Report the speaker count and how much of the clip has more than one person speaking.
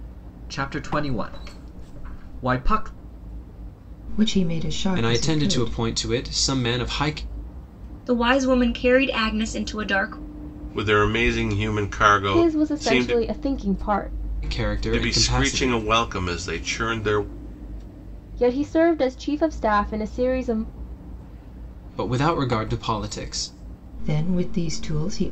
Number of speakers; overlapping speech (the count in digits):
6, about 11%